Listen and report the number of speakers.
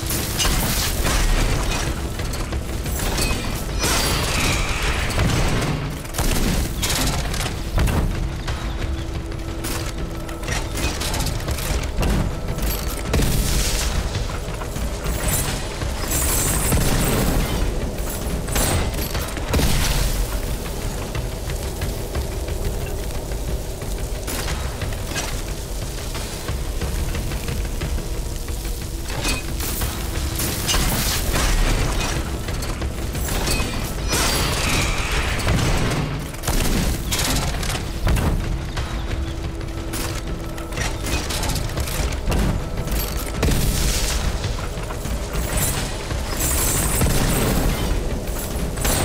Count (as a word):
zero